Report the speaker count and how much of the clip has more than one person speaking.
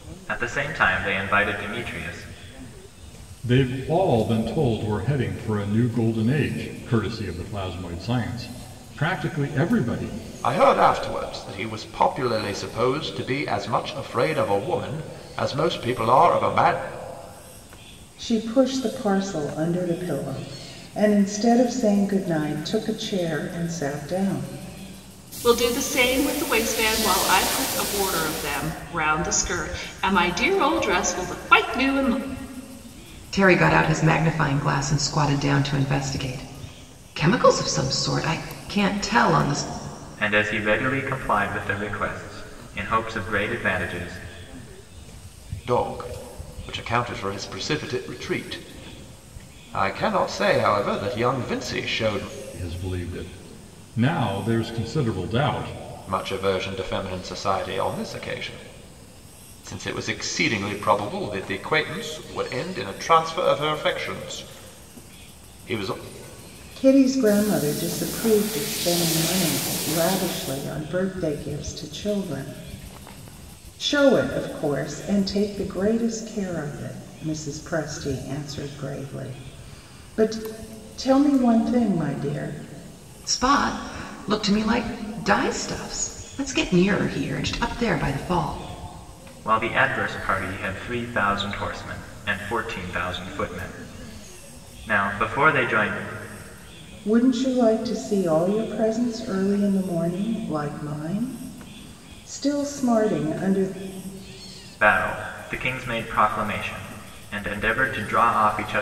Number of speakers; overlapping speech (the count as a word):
six, no overlap